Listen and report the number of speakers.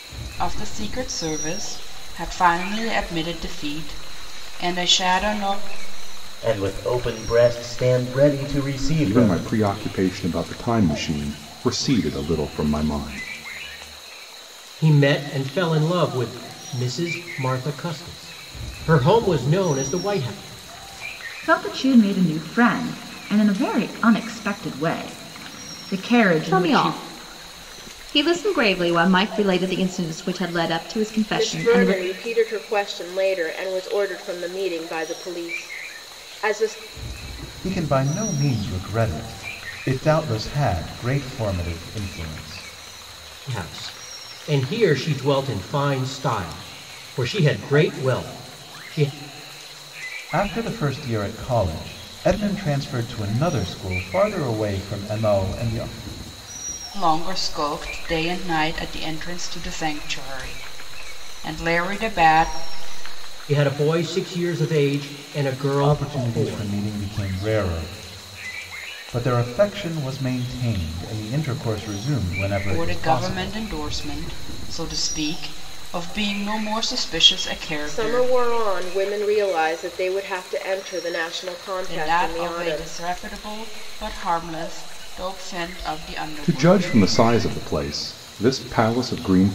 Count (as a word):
eight